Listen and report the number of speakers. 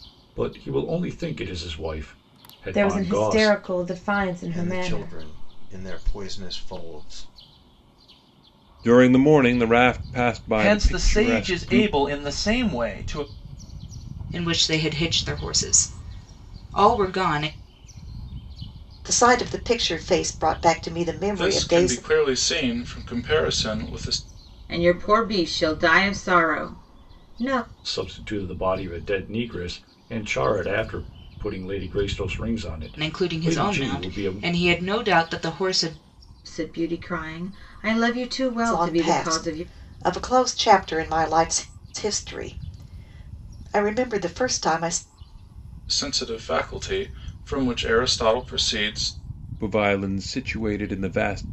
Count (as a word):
nine